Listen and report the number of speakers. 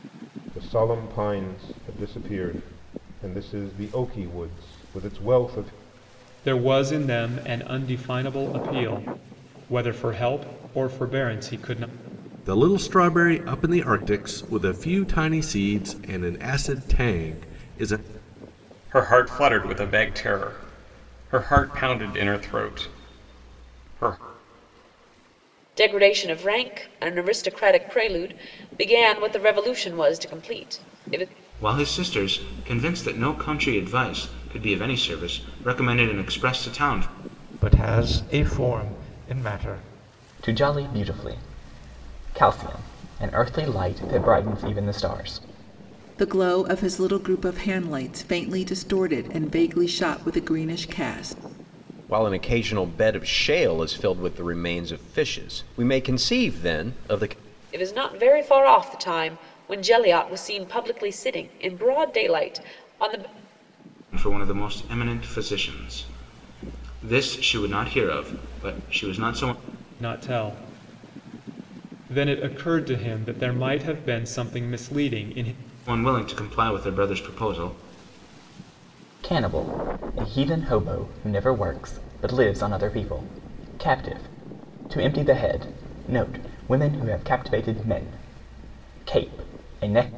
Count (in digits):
10